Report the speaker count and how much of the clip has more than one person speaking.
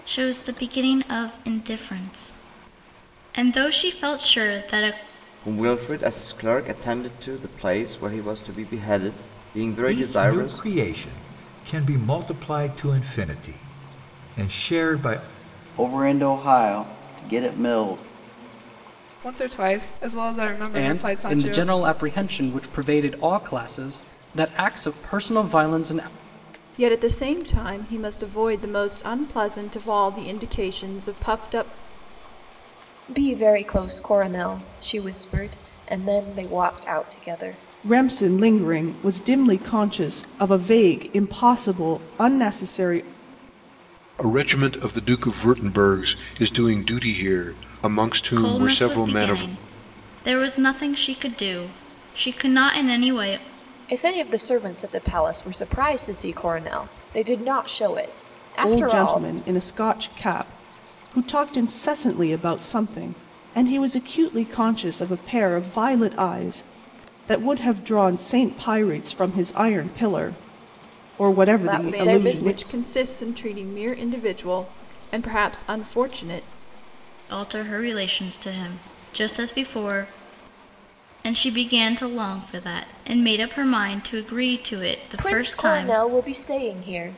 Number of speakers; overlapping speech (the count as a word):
ten, about 6%